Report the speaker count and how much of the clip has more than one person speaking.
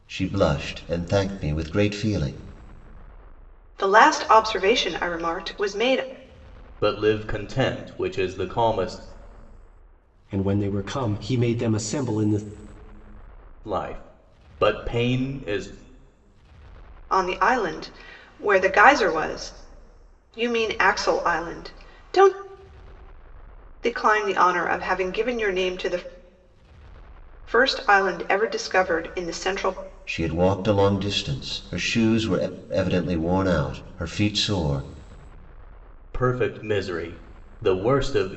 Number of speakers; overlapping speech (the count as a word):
four, no overlap